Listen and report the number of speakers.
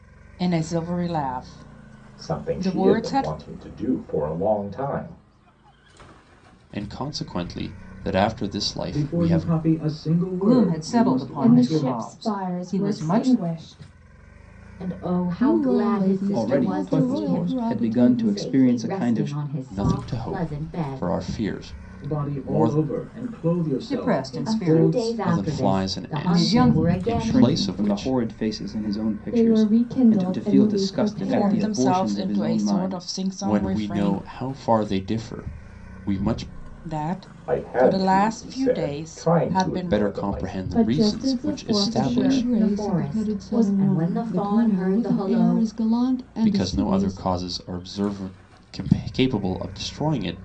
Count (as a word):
nine